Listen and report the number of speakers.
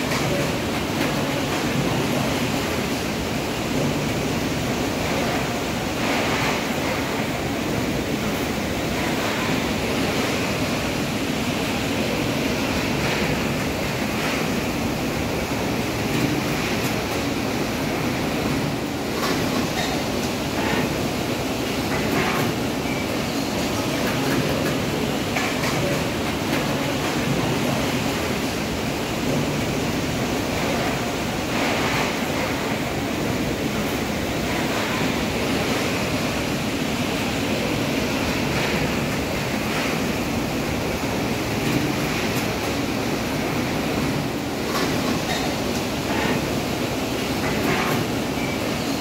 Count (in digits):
0